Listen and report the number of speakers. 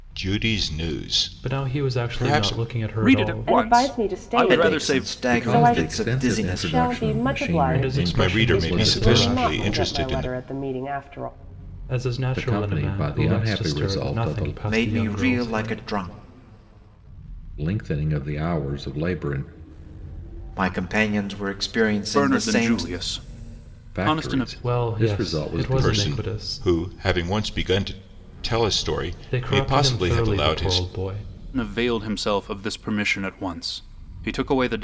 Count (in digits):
6